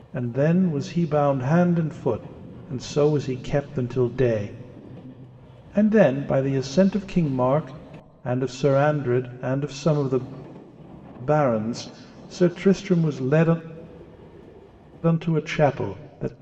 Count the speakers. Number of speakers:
one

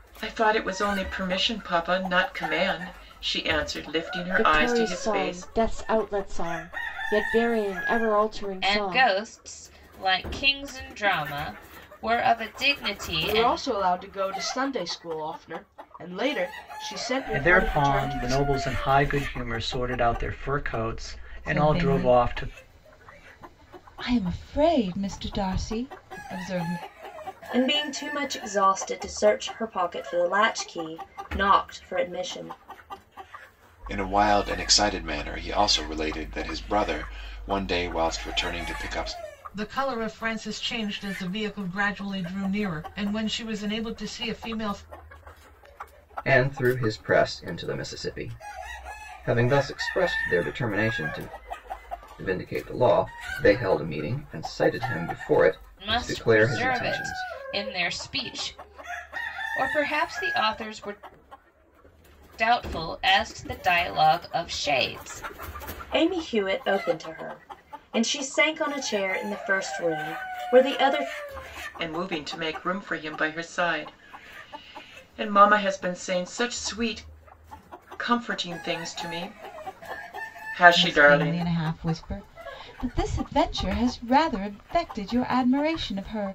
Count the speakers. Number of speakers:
ten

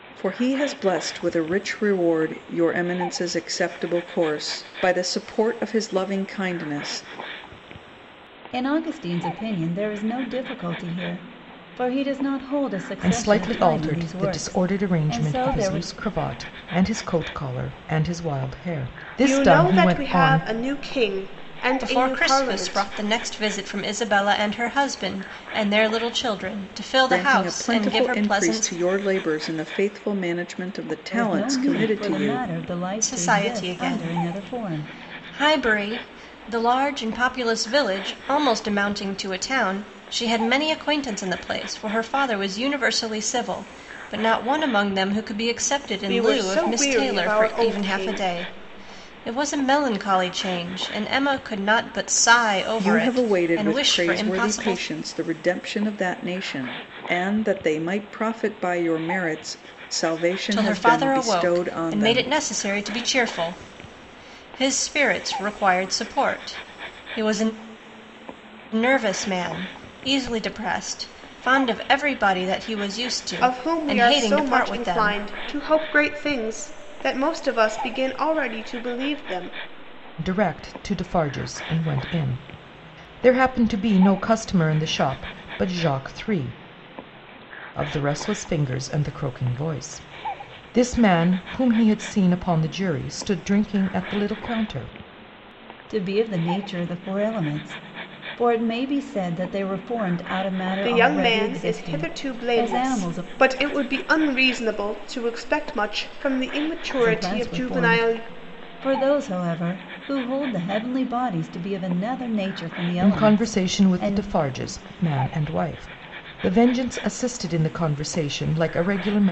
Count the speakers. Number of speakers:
five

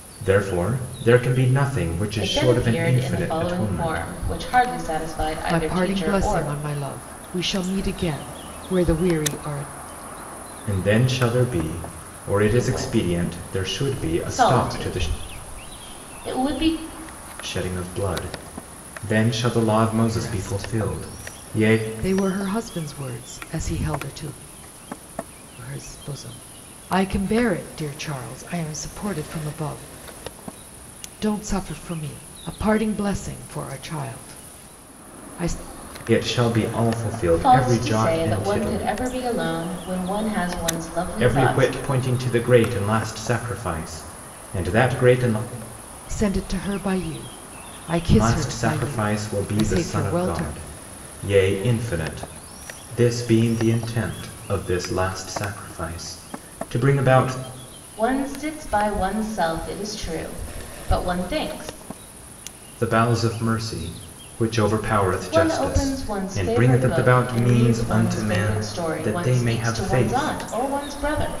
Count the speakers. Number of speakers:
three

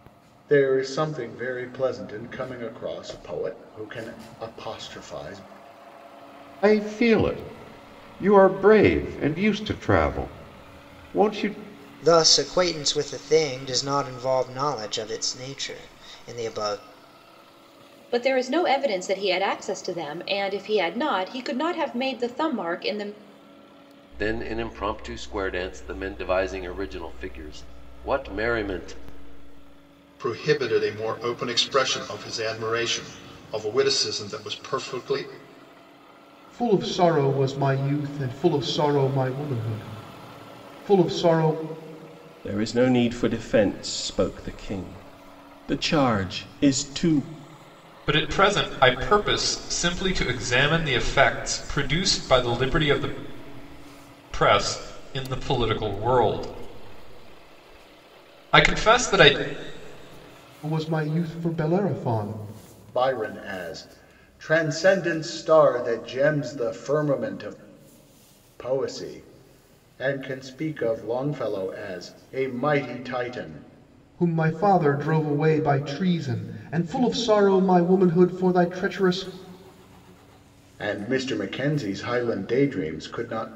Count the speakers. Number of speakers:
nine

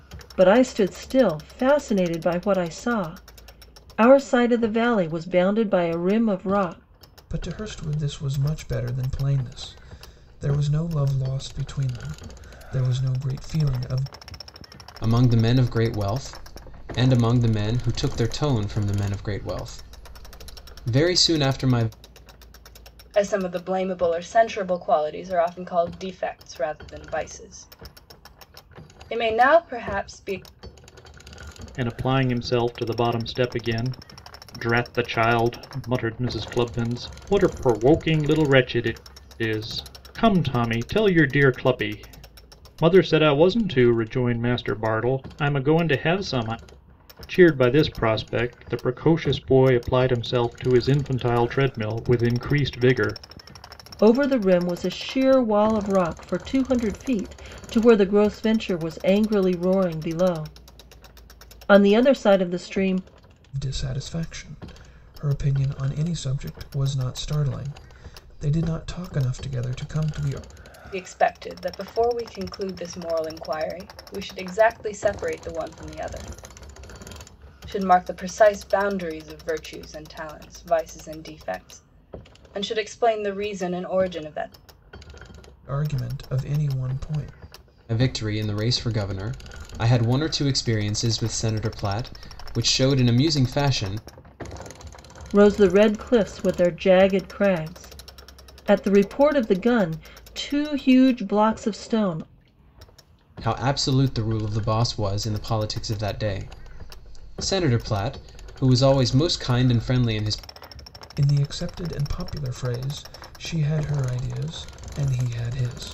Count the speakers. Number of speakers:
five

